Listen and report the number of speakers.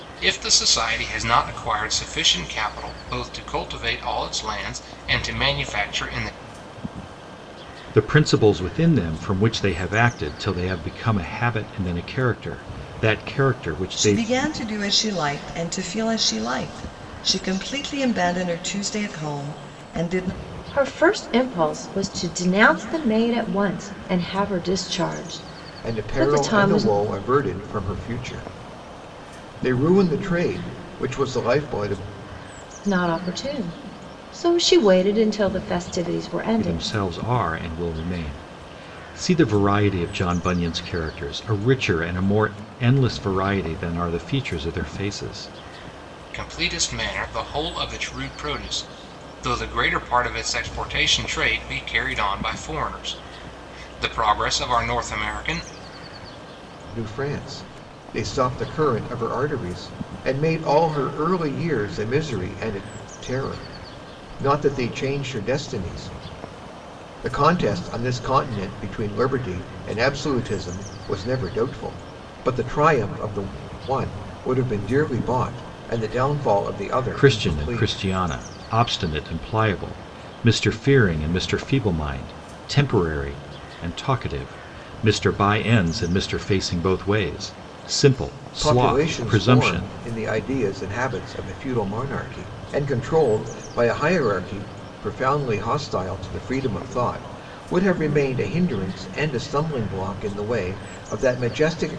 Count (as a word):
five